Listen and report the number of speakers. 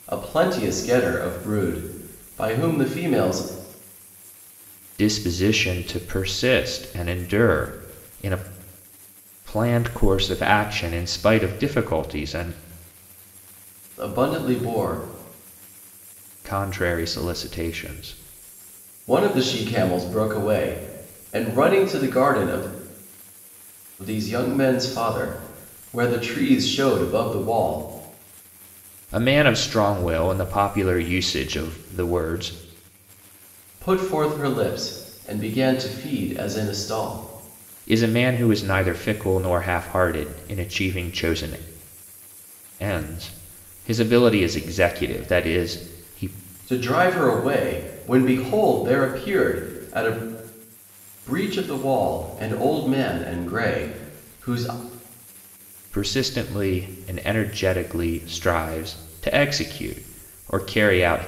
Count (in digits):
2